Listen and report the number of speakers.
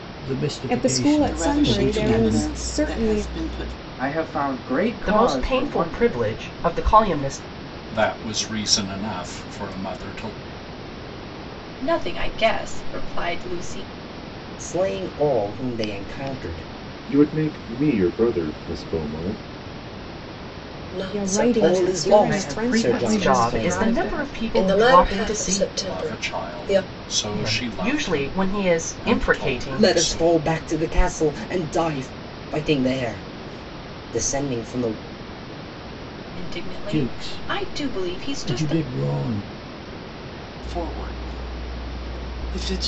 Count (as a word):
ten